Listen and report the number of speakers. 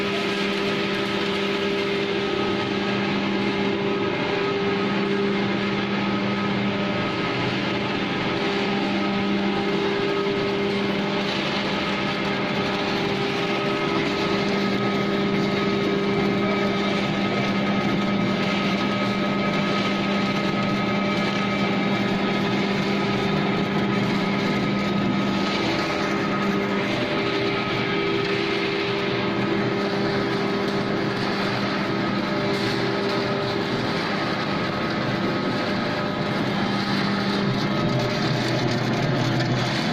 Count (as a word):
zero